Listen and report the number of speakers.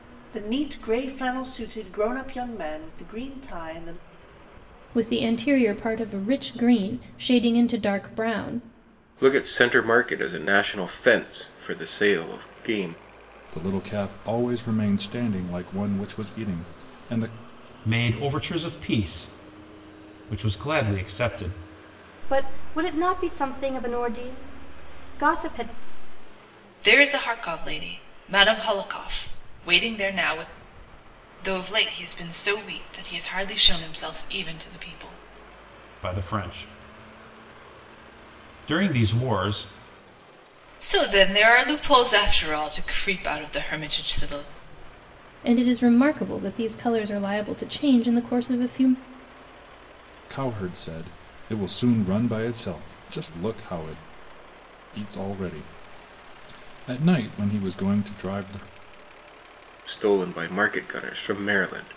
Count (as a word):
seven